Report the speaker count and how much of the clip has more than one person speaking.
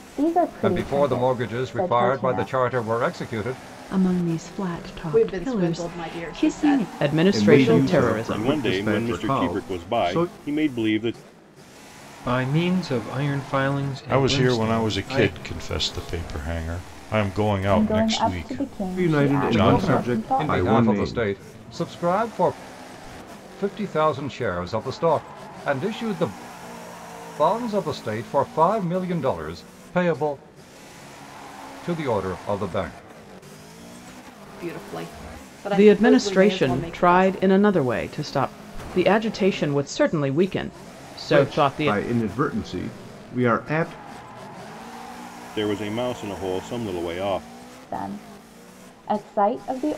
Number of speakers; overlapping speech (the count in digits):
9, about 29%